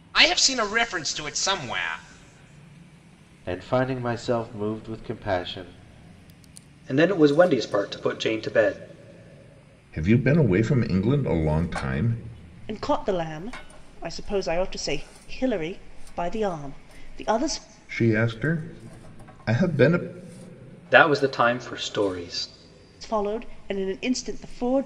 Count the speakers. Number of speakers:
5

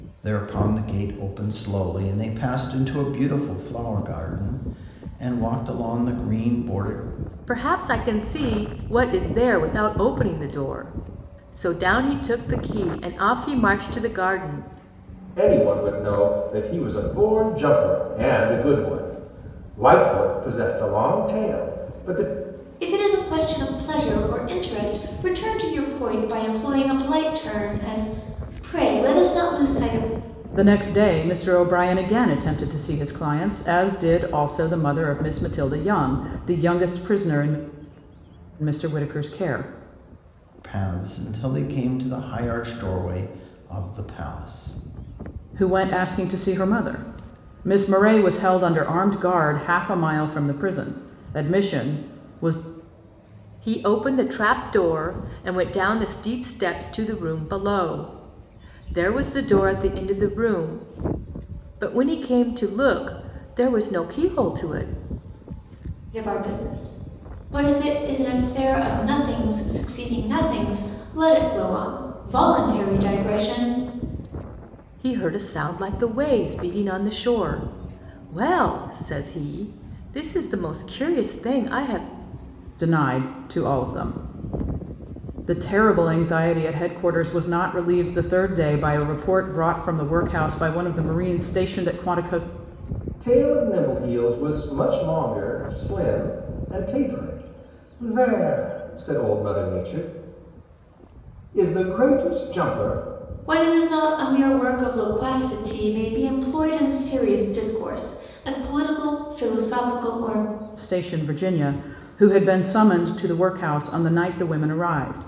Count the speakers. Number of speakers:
5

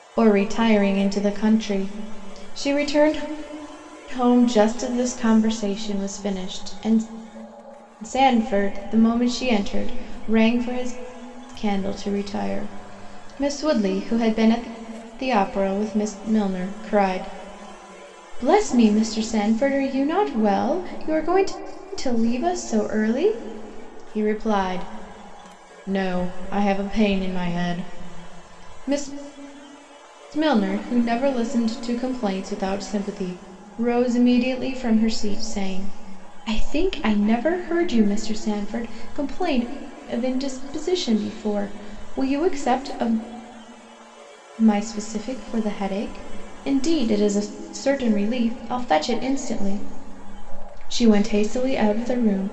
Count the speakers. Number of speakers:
1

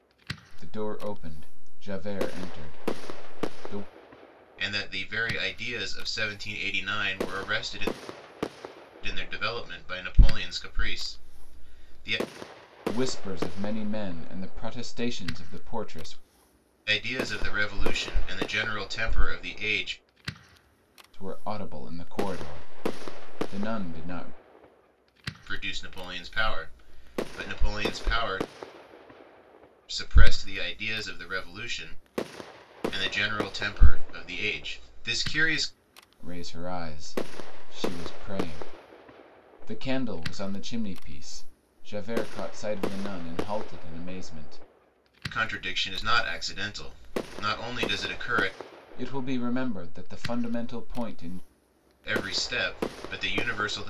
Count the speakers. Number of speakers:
2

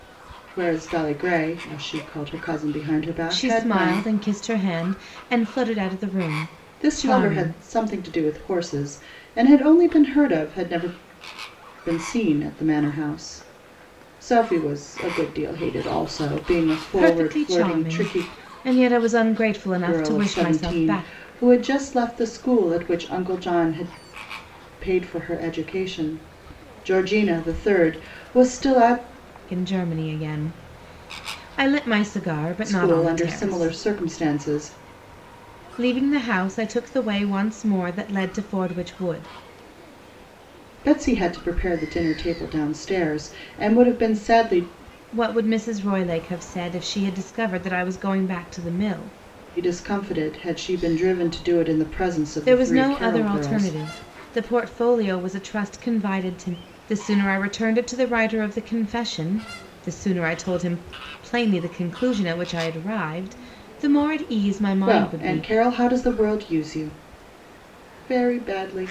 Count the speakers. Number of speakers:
2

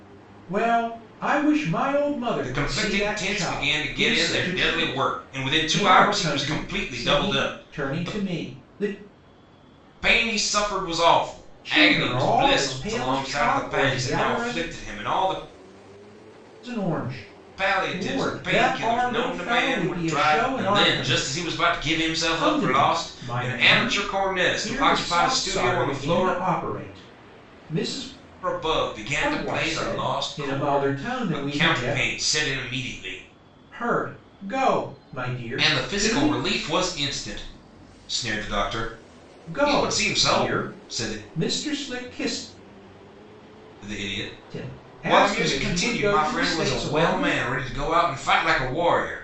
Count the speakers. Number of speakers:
2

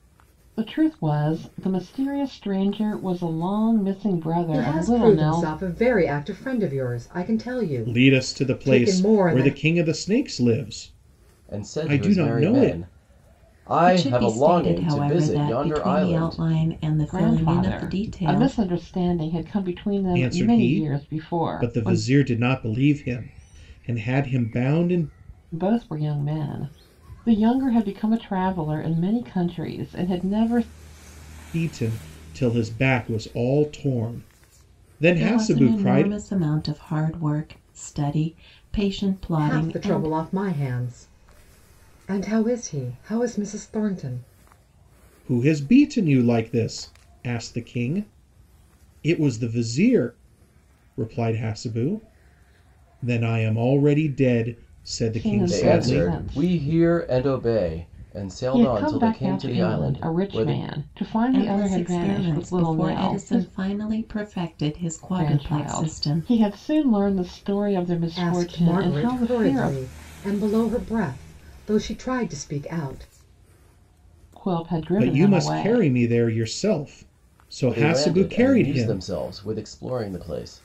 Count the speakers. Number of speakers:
5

